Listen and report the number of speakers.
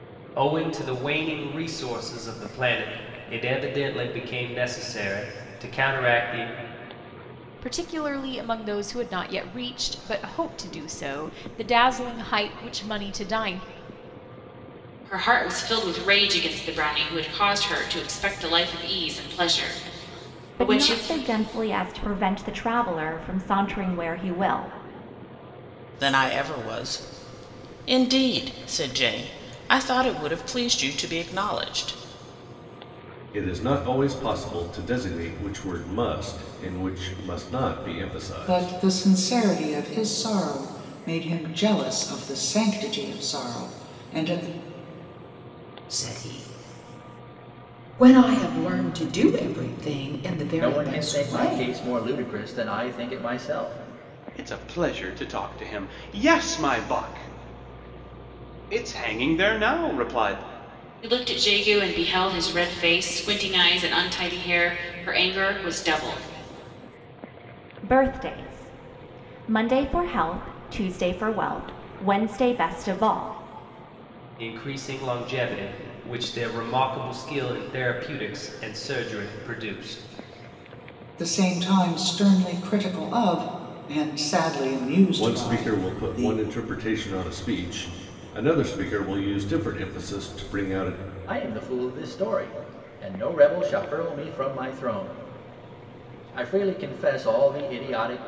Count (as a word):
ten